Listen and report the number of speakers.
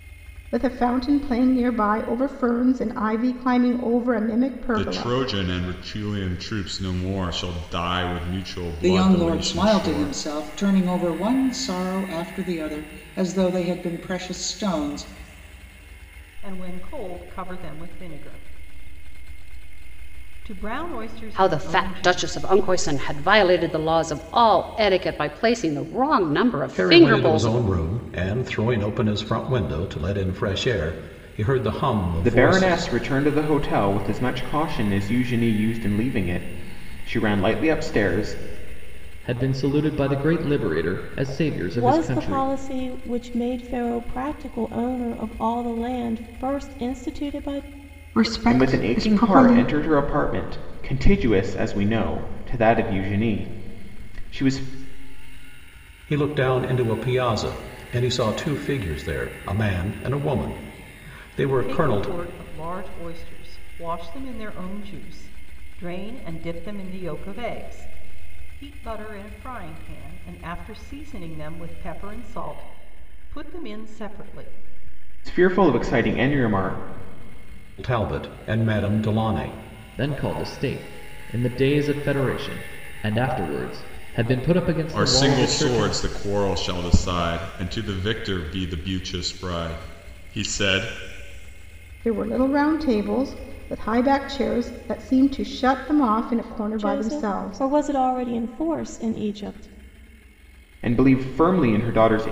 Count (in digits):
10